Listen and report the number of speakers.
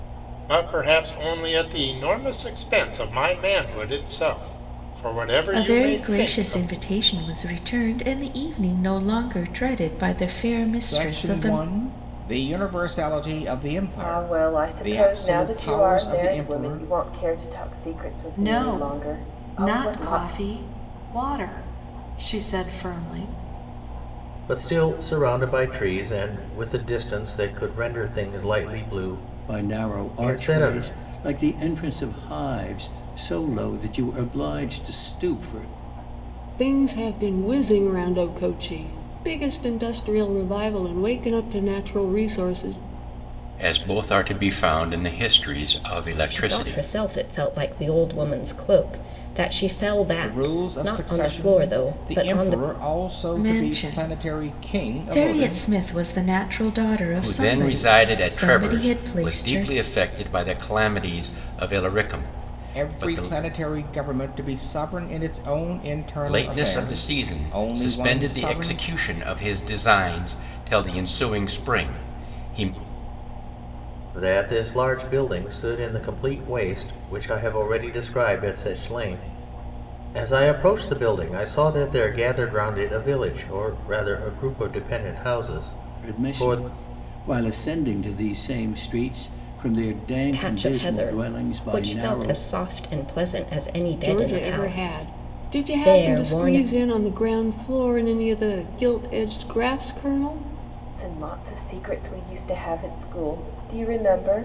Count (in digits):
10